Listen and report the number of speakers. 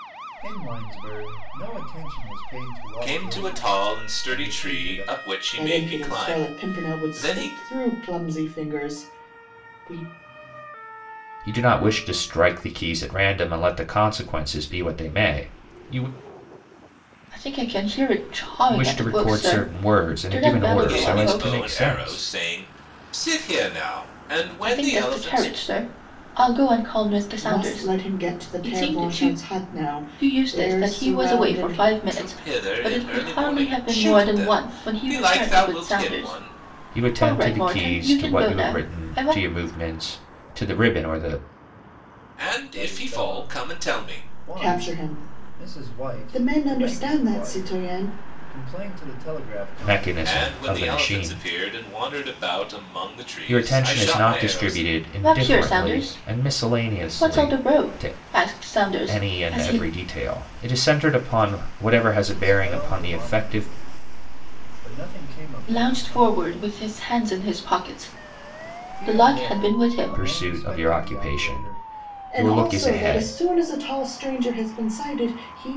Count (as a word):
five